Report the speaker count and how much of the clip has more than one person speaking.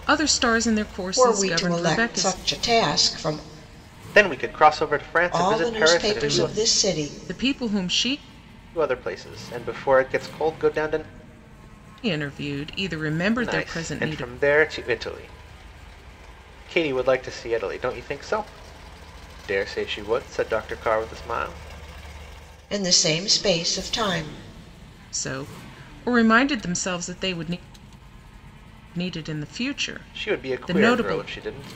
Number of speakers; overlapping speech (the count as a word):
three, about 17%